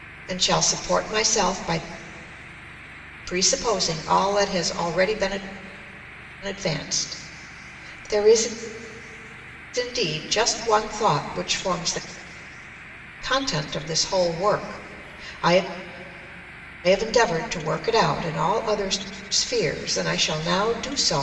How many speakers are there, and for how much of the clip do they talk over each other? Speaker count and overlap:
1, no overlap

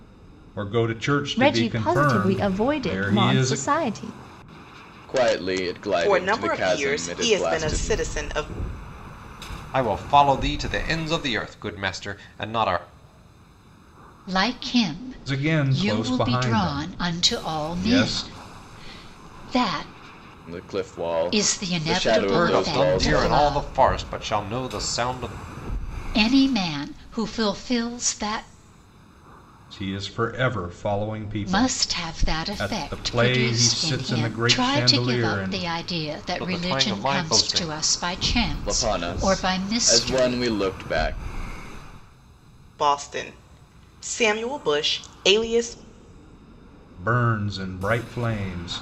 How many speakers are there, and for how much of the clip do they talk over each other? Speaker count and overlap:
6, about 35%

